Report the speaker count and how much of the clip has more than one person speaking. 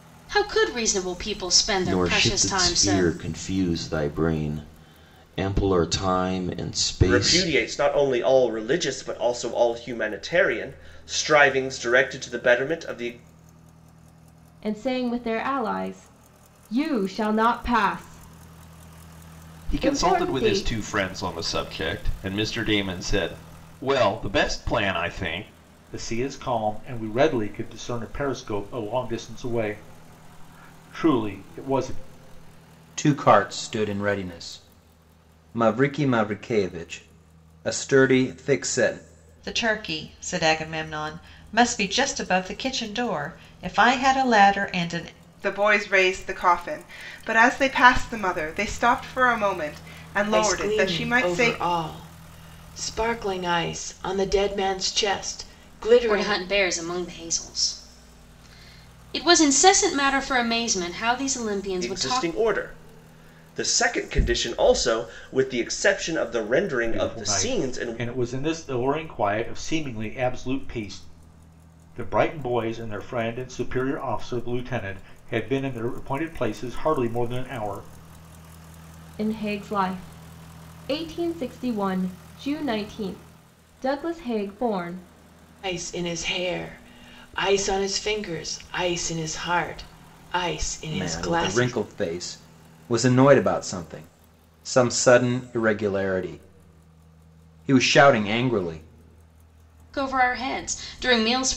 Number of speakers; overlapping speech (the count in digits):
10, about 7%